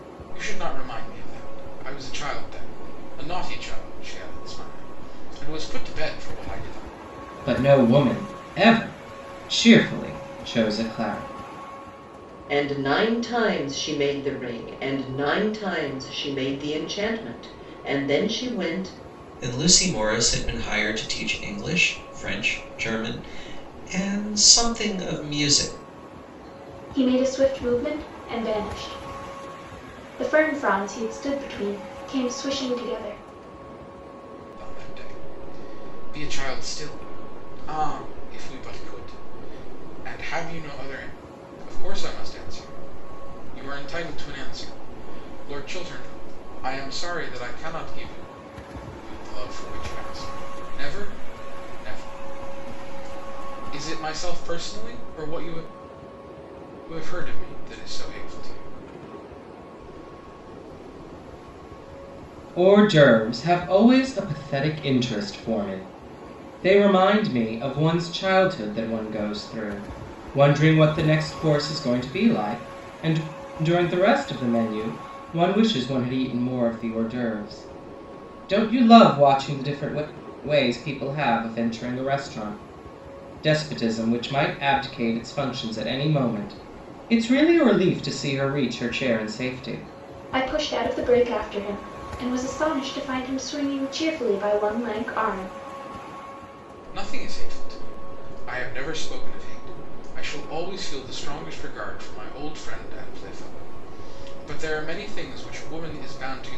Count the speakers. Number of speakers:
5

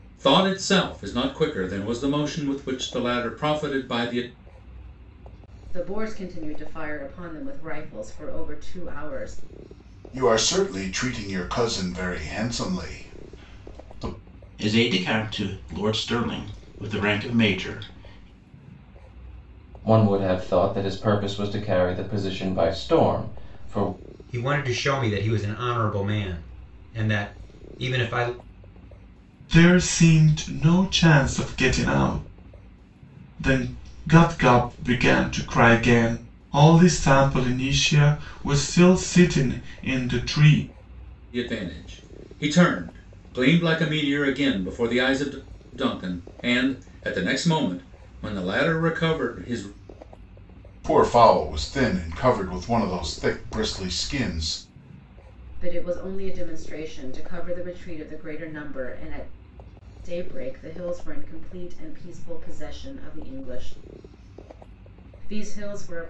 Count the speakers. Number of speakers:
7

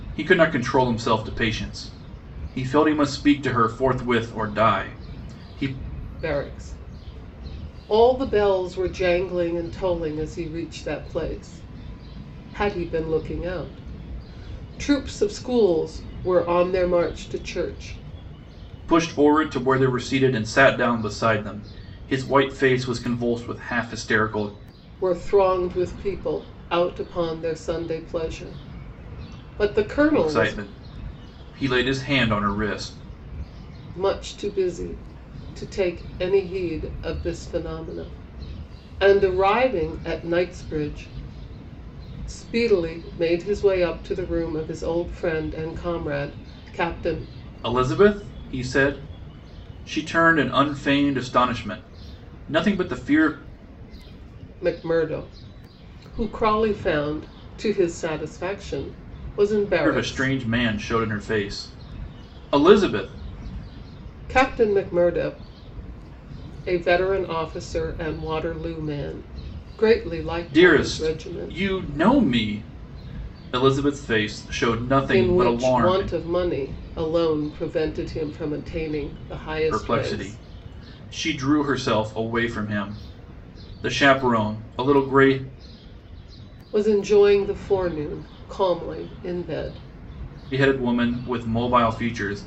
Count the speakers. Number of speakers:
2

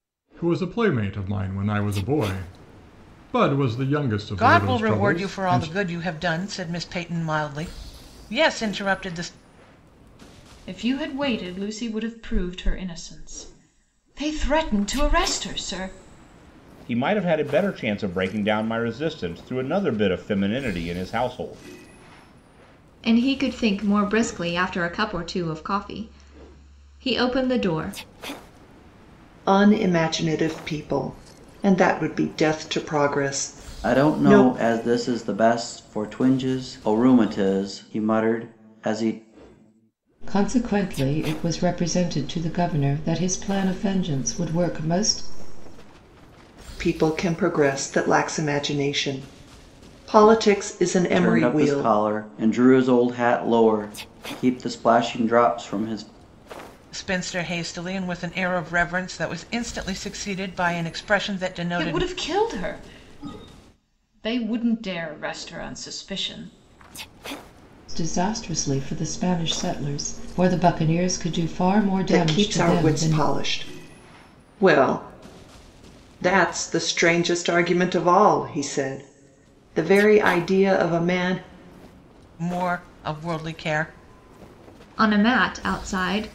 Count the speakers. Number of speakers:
8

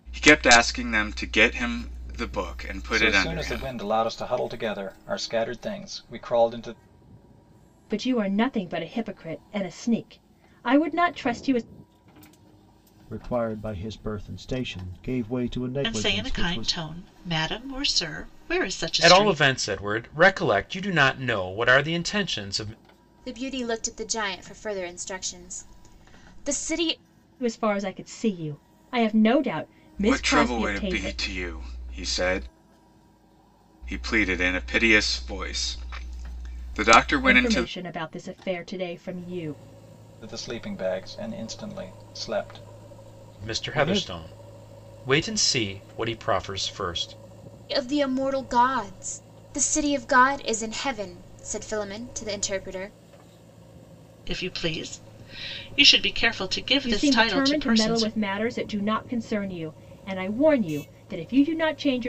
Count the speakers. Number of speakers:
7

